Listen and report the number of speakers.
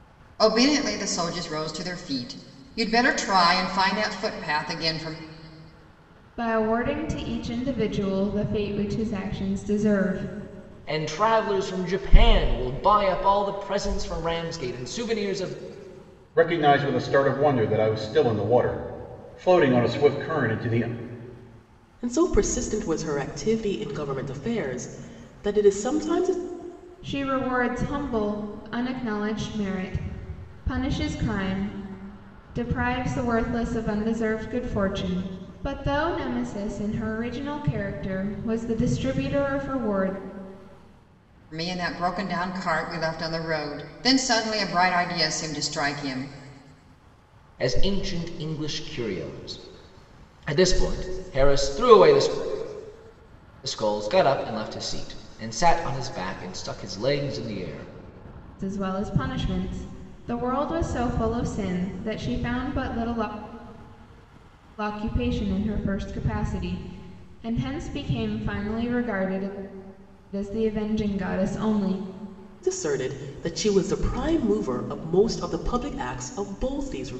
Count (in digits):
5